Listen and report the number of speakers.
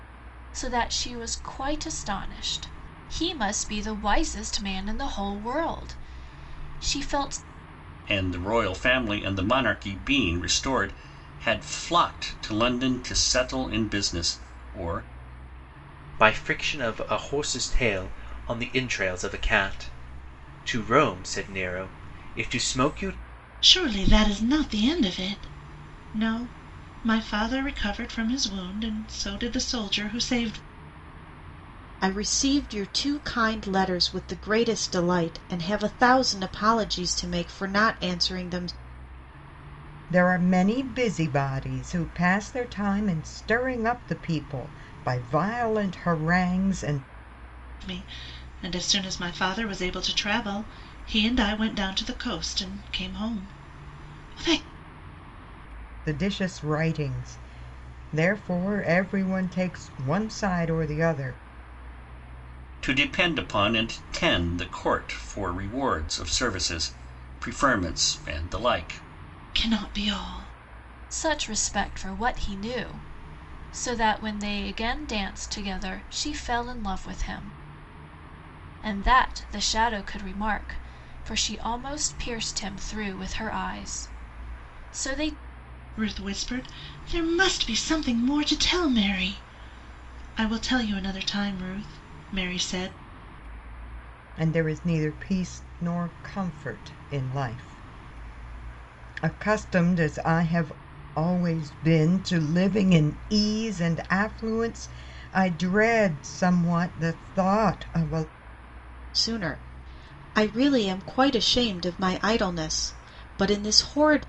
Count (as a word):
six